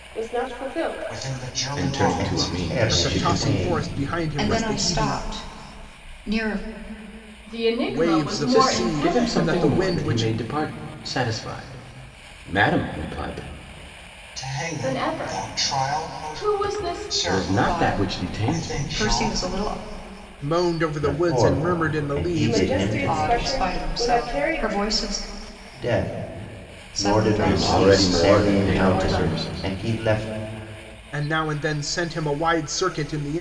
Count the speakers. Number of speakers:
seven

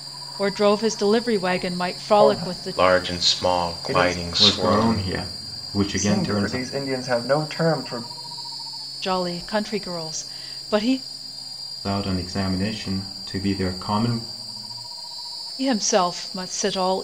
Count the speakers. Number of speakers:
four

